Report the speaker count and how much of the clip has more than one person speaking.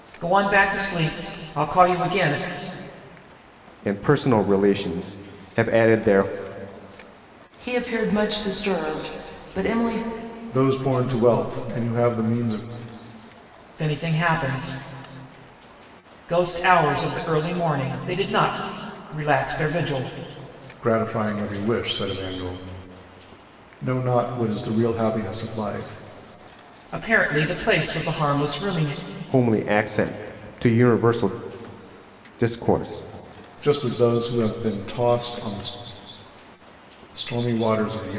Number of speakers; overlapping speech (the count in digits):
4, no overlap